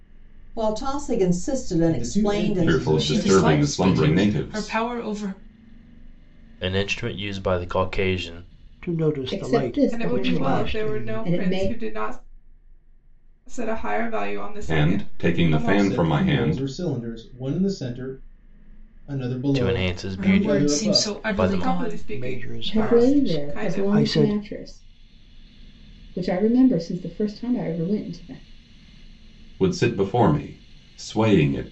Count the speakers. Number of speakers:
eight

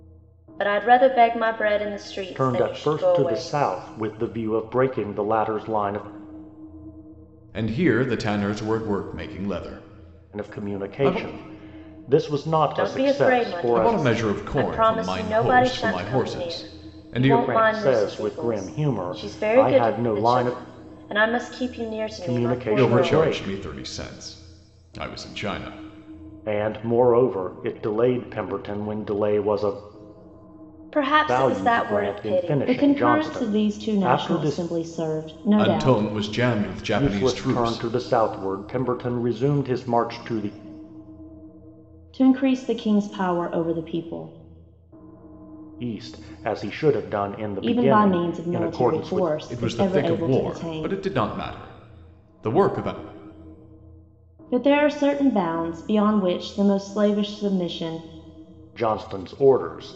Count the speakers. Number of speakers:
three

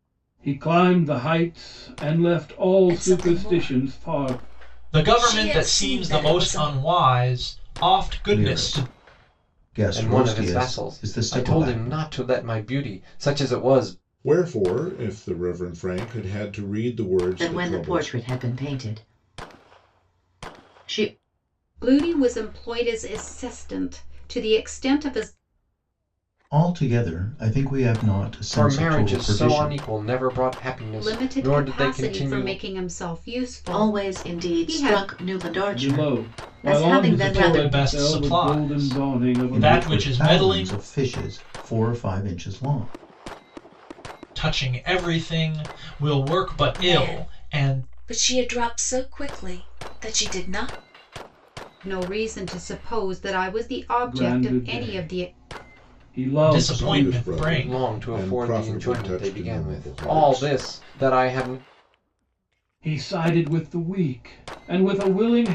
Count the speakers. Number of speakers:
eight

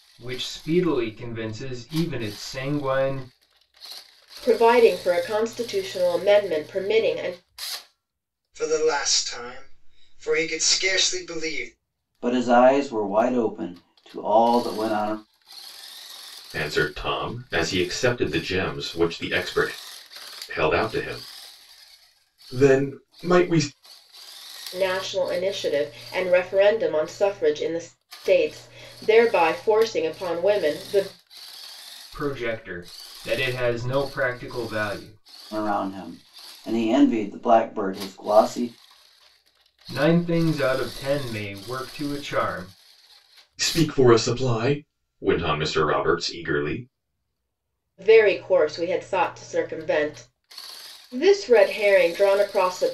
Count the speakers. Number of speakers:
five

